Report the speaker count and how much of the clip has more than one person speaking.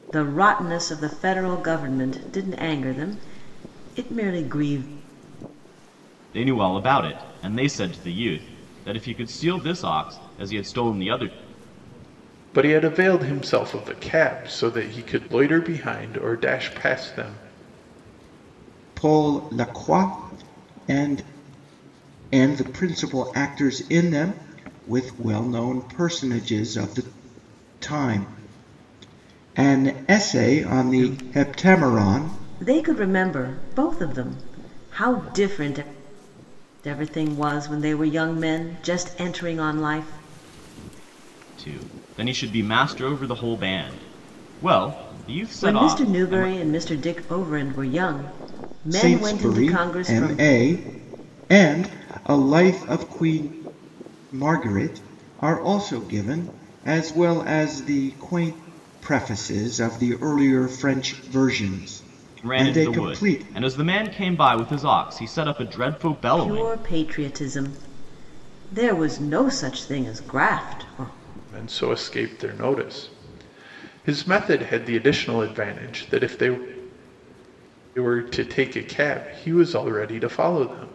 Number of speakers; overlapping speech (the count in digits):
4, about 7%